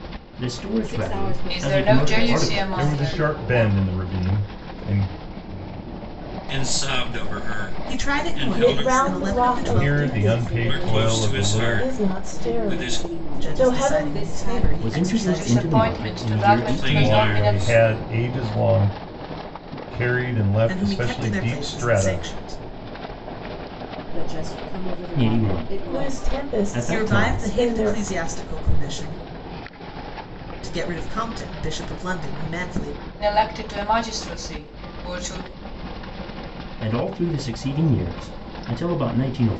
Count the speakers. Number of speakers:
7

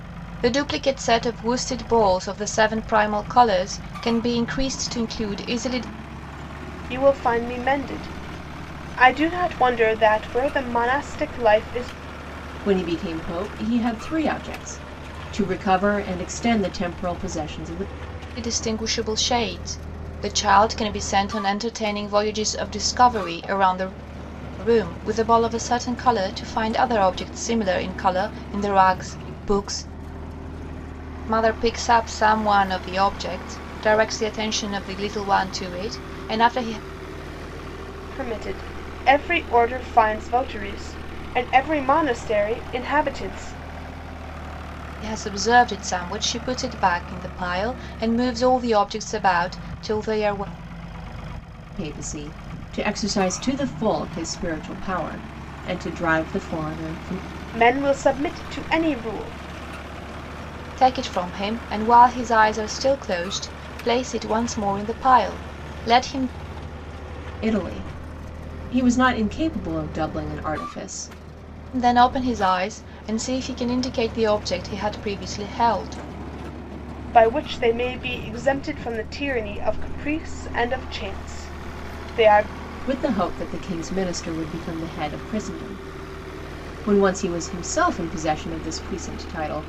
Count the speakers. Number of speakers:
3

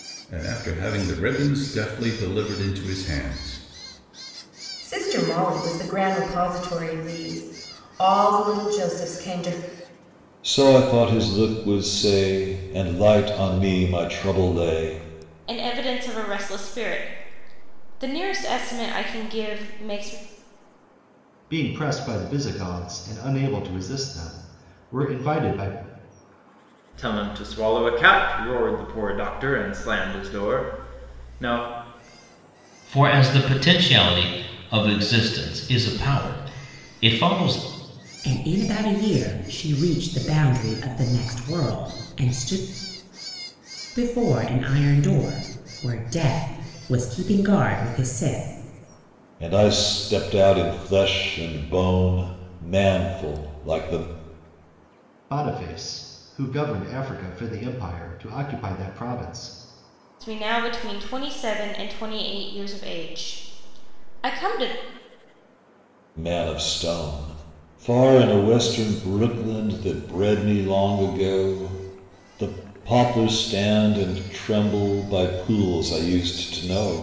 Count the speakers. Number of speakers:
8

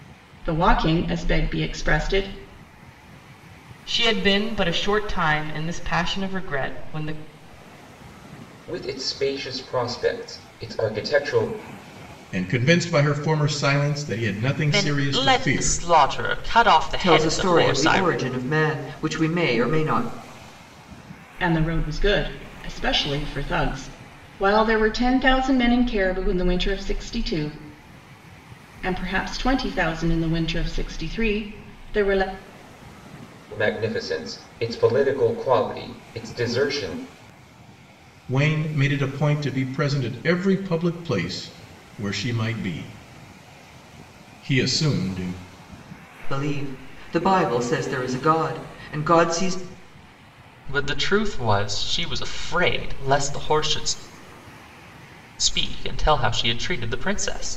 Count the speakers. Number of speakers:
6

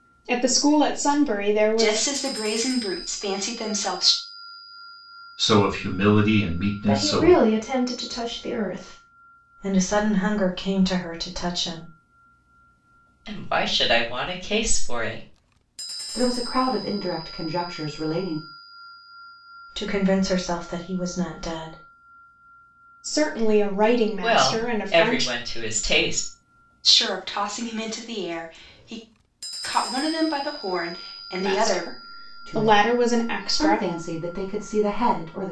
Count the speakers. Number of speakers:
7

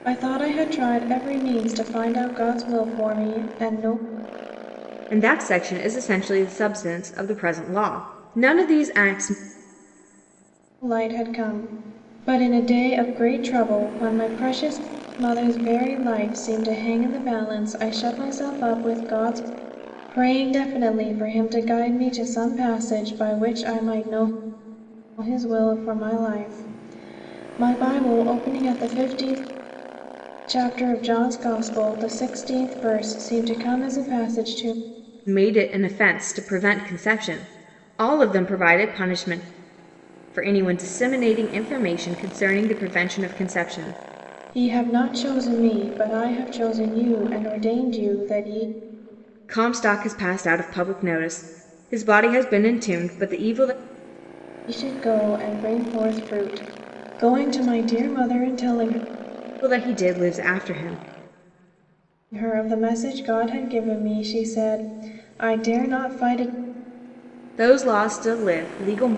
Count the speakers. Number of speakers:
2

